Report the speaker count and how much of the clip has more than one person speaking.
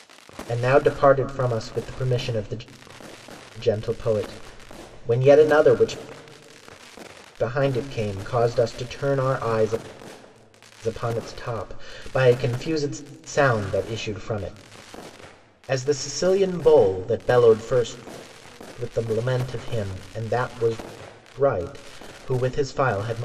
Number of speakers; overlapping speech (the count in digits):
1, no overlap